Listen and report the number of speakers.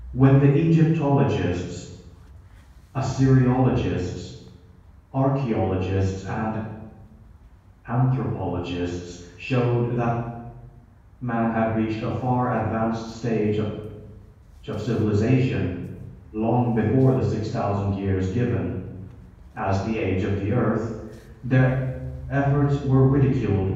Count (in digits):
1